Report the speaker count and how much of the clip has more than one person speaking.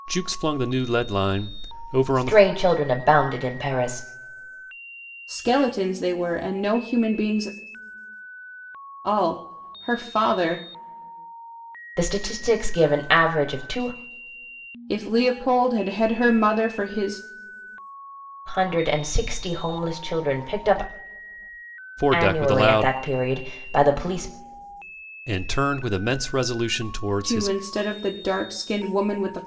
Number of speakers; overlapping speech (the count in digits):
3, about 5%